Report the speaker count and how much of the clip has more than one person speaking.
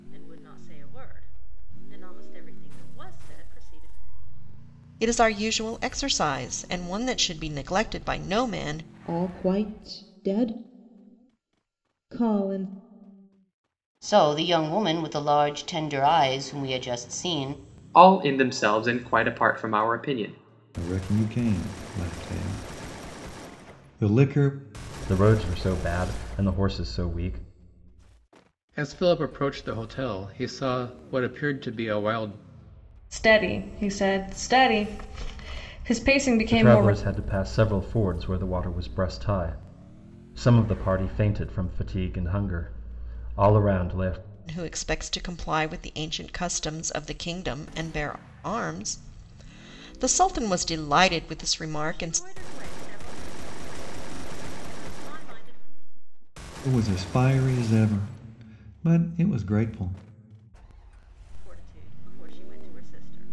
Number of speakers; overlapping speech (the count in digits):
9, about 2%